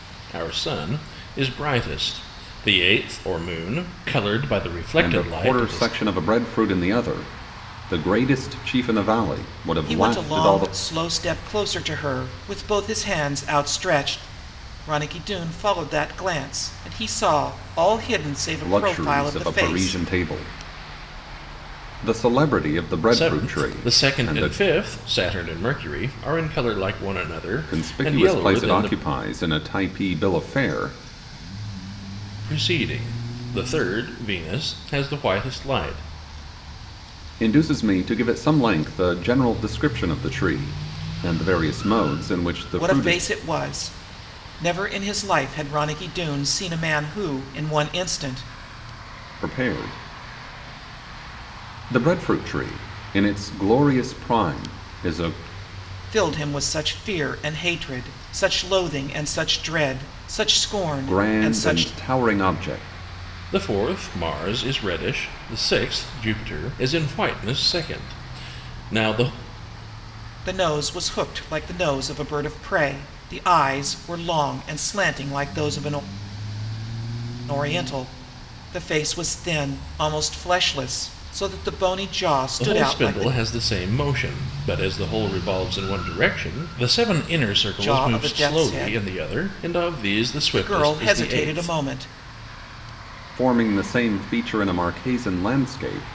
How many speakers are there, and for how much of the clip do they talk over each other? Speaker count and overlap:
three, about 11%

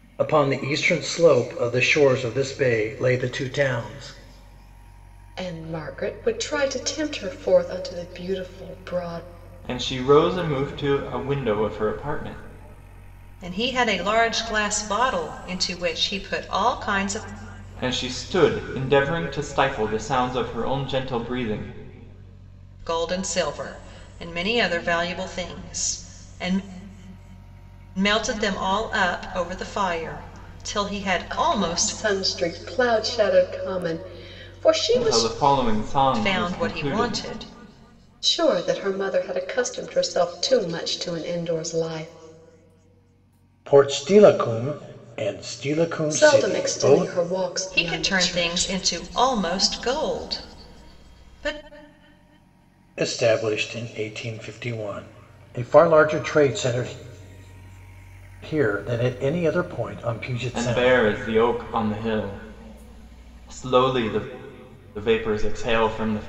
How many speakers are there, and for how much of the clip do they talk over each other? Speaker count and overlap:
four, about 7%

